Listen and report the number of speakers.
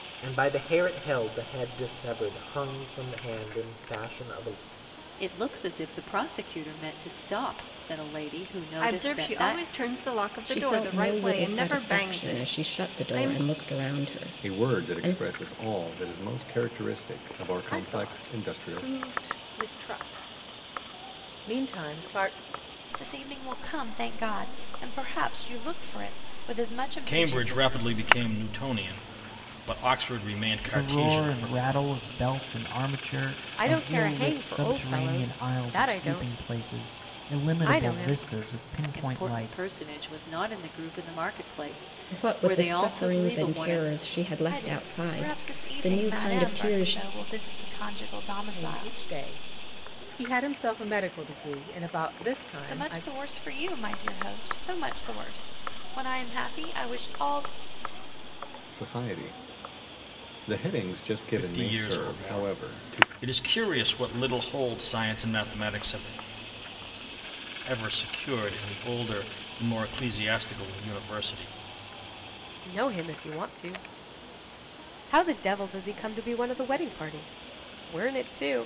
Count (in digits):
10